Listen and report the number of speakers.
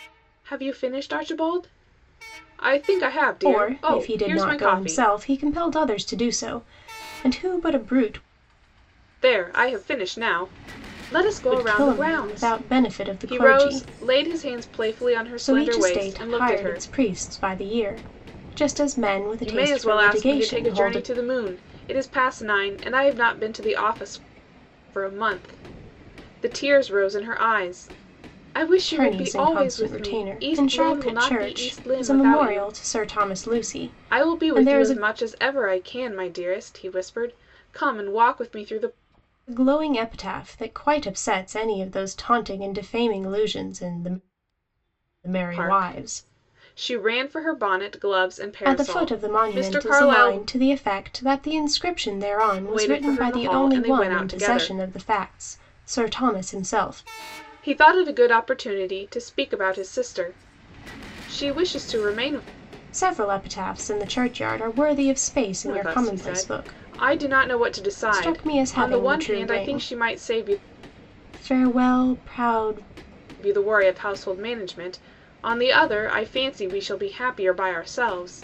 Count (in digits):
2